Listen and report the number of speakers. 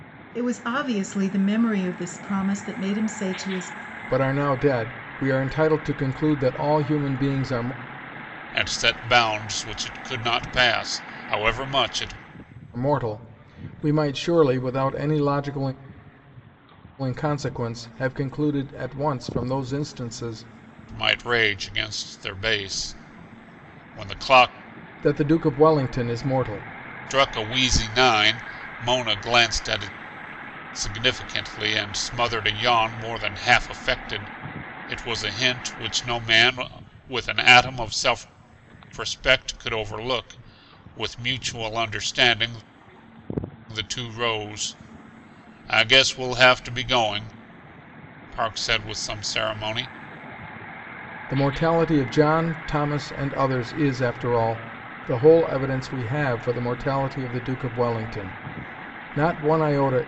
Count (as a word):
three